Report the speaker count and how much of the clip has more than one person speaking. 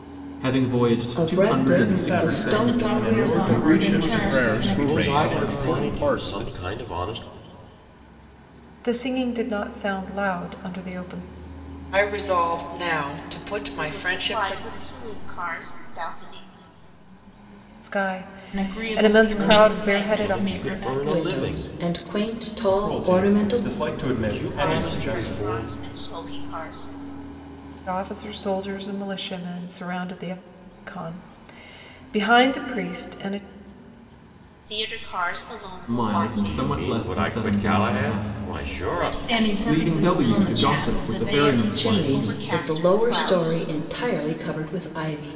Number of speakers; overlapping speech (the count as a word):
ten, about 44%